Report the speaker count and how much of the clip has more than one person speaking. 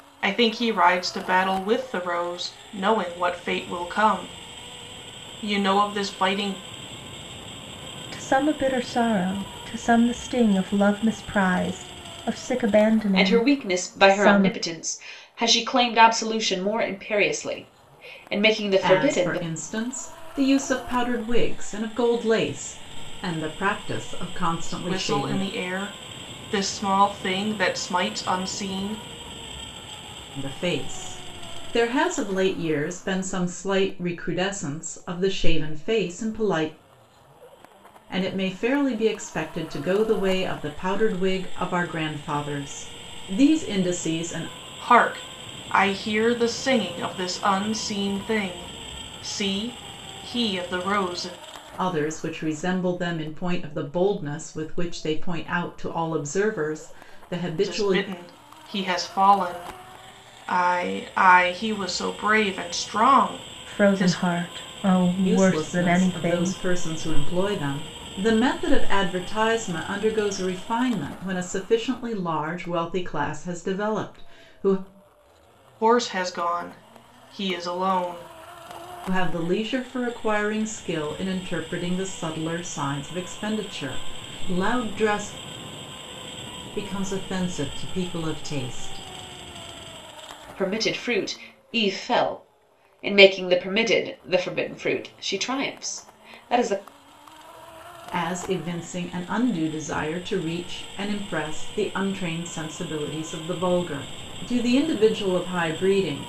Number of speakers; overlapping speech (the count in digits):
4, about 5%